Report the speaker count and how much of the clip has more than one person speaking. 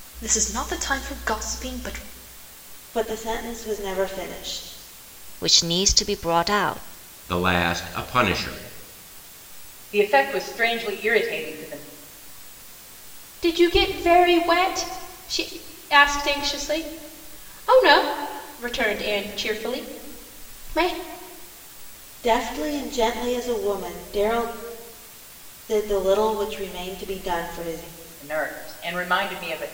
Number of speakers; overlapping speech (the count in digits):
6, no overlap